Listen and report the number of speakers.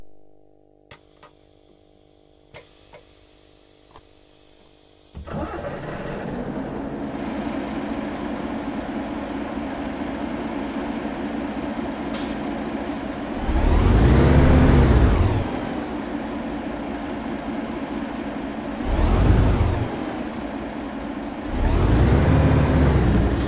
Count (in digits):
0